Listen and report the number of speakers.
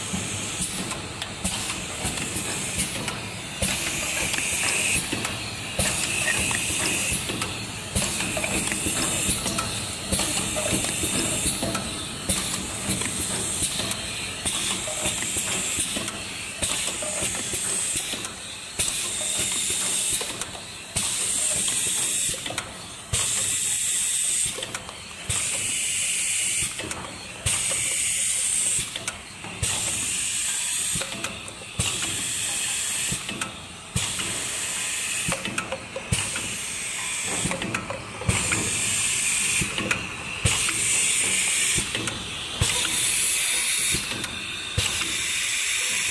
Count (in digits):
0